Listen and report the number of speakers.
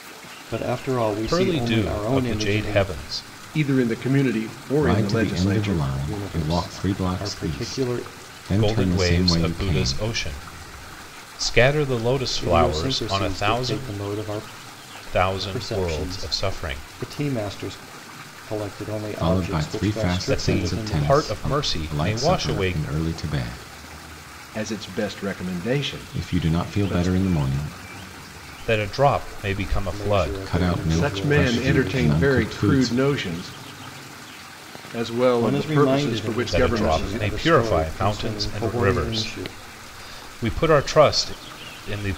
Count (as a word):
four